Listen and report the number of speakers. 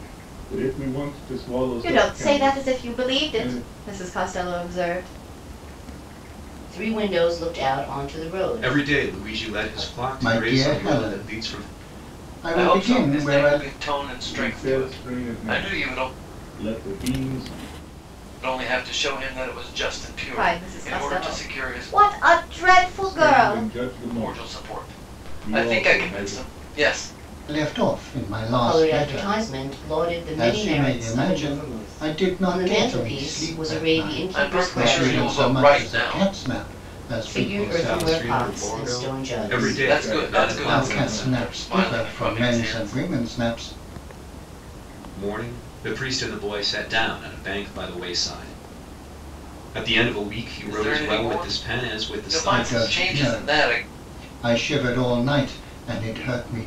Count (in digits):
6